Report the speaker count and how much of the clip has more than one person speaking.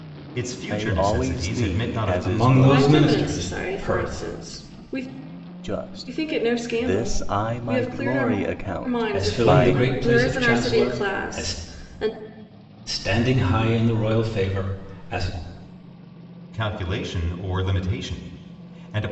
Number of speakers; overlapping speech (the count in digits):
4, about 45%